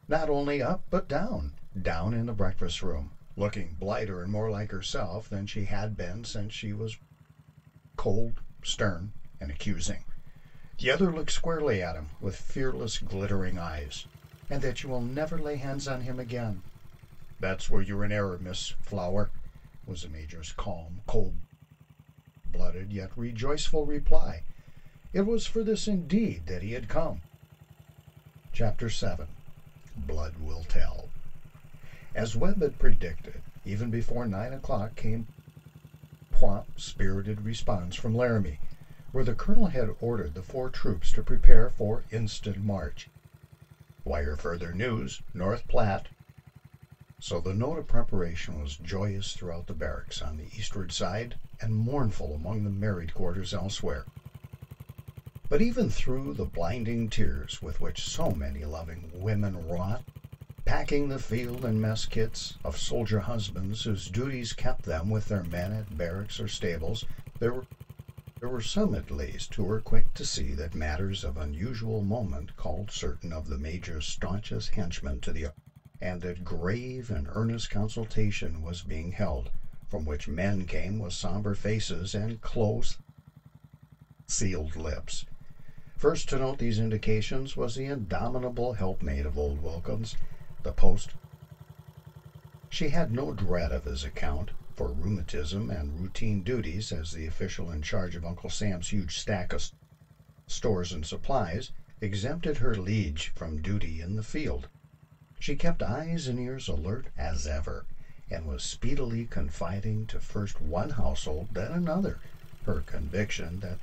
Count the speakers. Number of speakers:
1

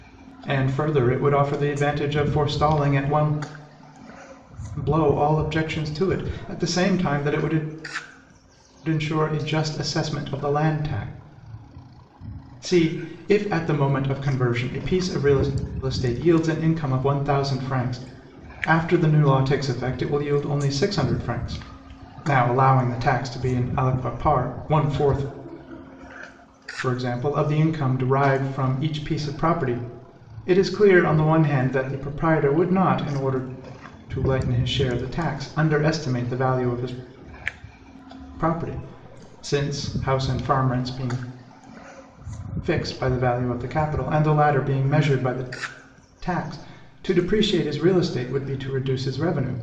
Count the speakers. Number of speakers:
1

